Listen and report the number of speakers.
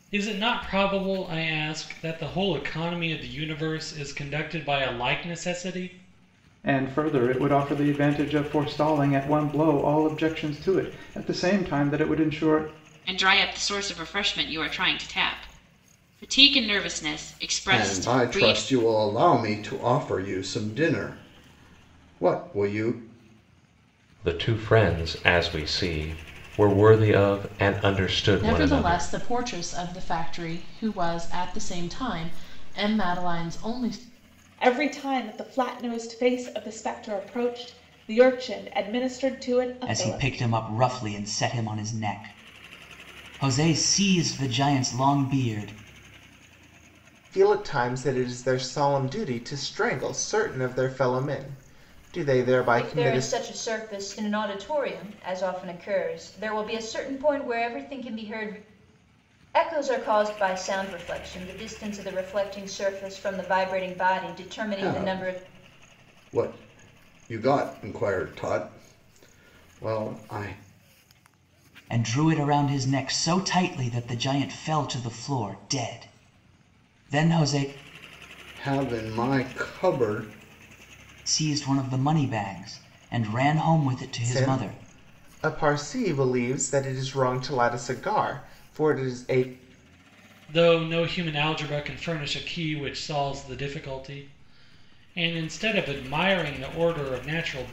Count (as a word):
ten